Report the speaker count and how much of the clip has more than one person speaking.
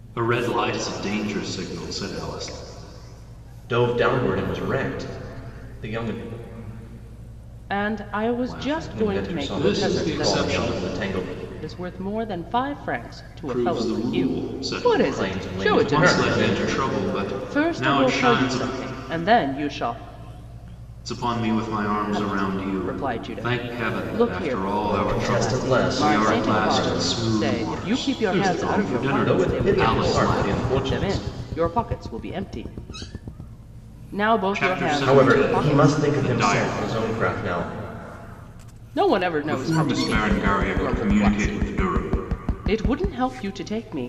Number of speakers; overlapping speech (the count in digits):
3, about 46%